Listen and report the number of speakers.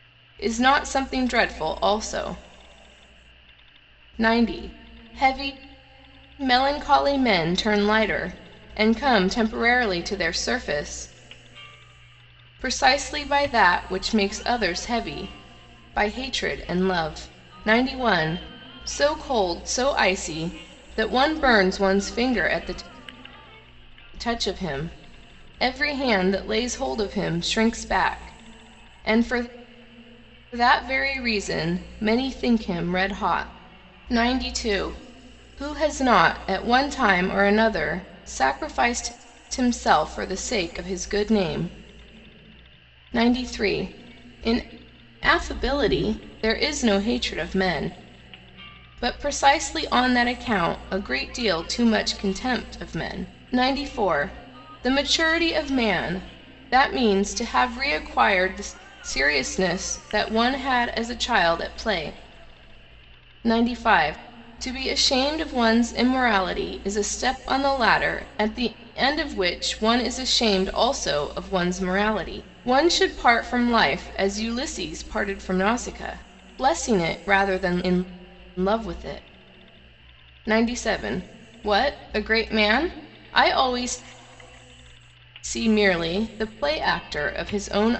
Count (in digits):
1